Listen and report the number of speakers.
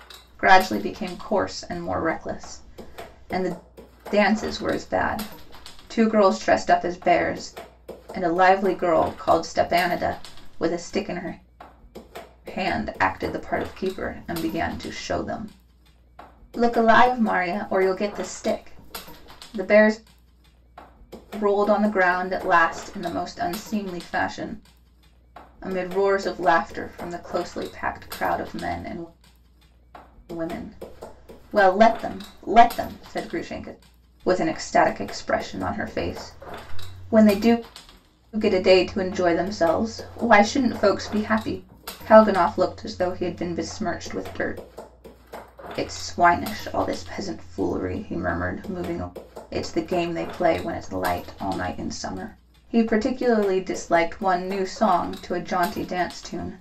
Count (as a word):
one